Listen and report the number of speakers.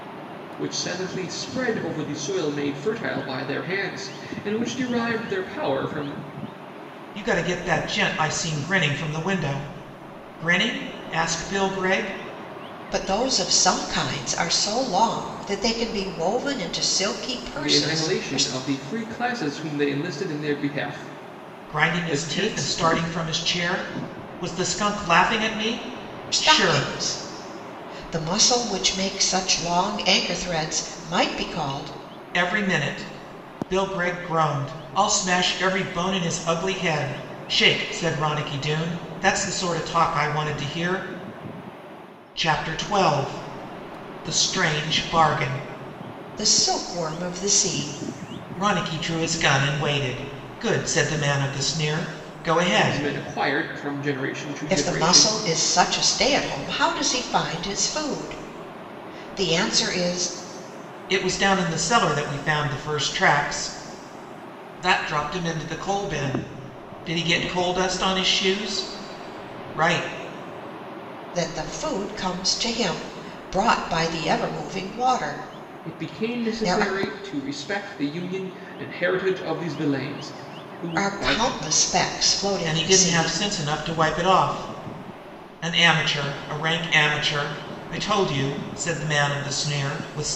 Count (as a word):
three